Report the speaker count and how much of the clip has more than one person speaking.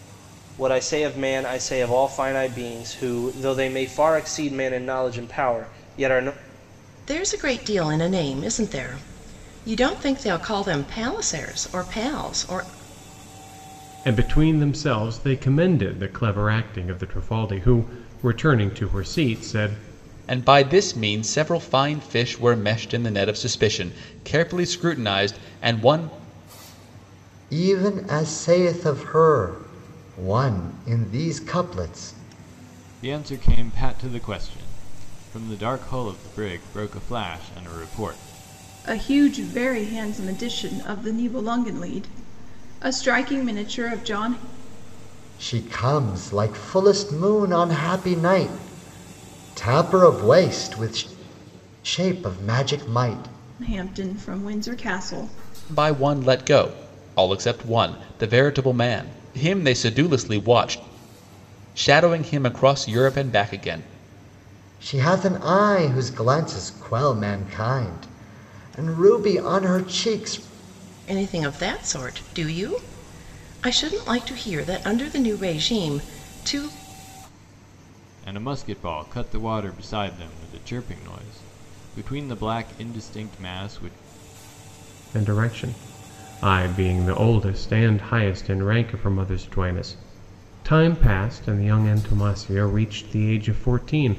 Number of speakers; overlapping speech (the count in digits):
7, no overlap